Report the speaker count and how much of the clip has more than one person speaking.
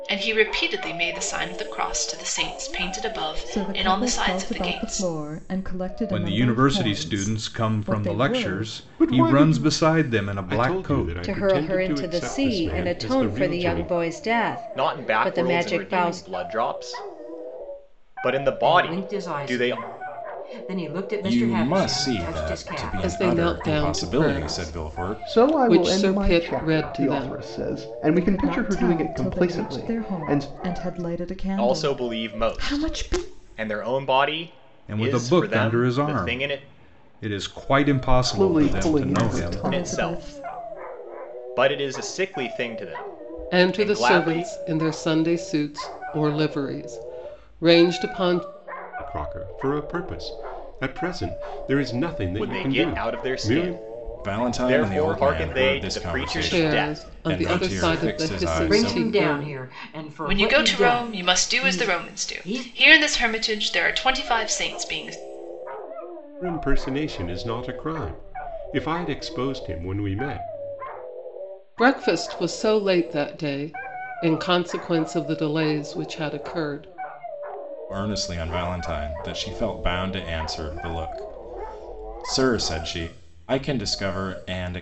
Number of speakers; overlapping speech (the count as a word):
ten, about 43%